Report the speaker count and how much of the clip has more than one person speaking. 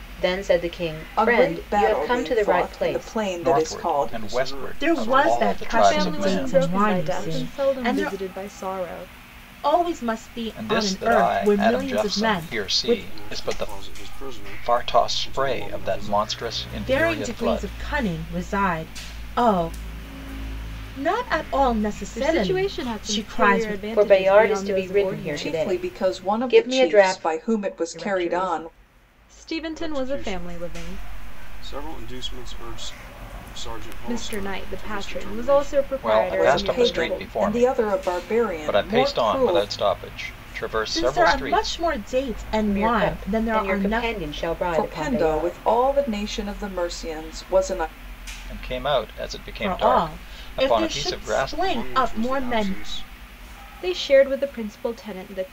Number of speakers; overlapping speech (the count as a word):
six, about 57%